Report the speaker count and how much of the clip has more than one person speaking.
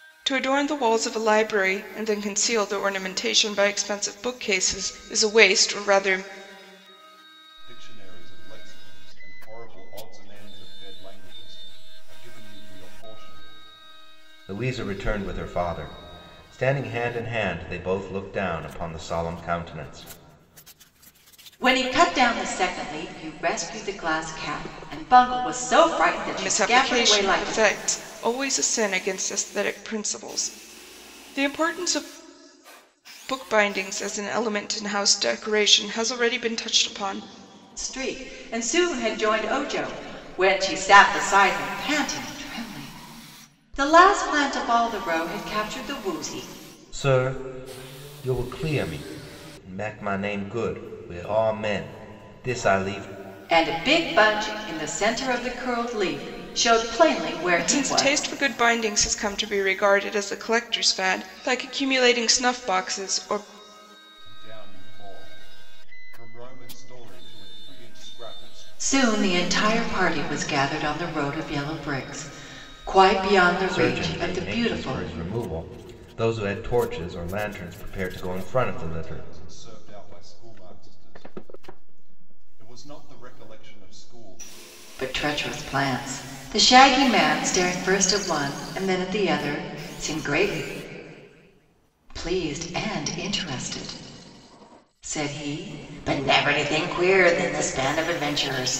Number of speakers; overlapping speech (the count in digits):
4, about 6%